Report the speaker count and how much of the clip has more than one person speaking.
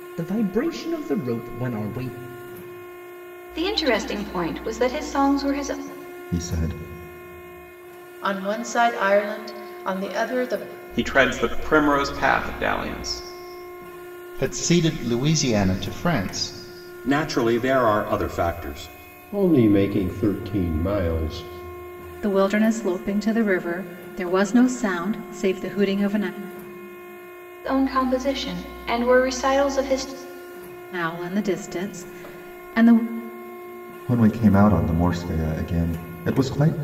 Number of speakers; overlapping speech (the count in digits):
9, no overlap